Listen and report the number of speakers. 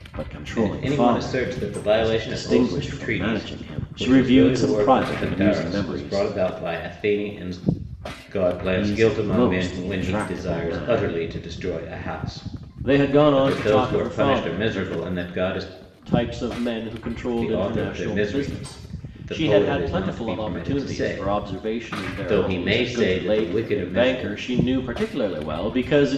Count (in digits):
2